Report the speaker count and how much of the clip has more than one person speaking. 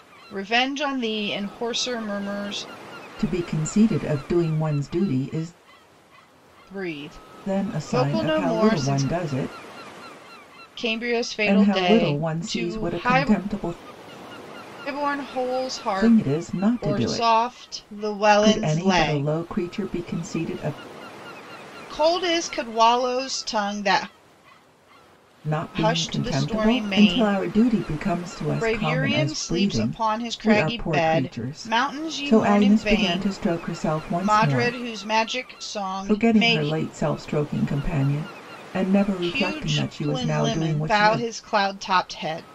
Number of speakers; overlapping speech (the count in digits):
2, about 36%